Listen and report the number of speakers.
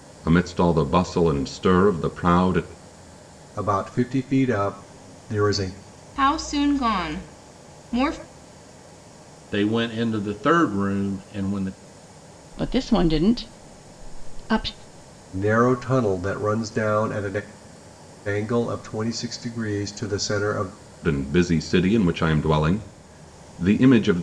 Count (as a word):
five